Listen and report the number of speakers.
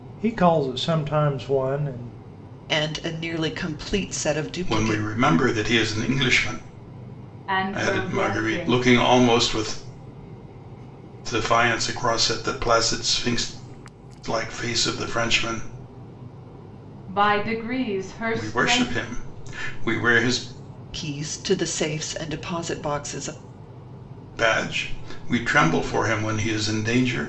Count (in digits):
4